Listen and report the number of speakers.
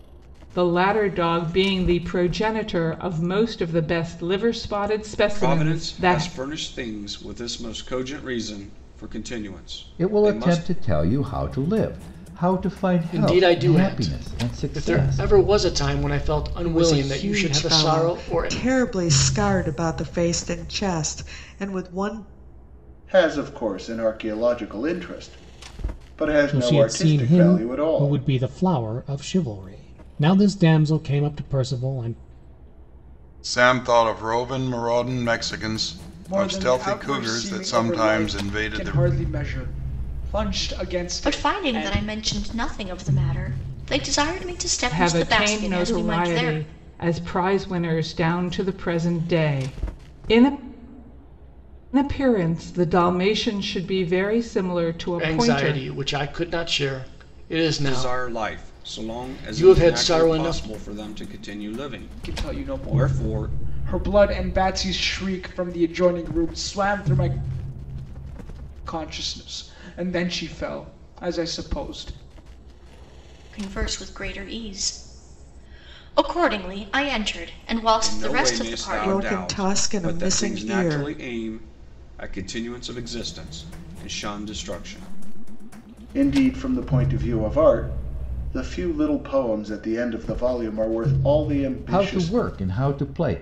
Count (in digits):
10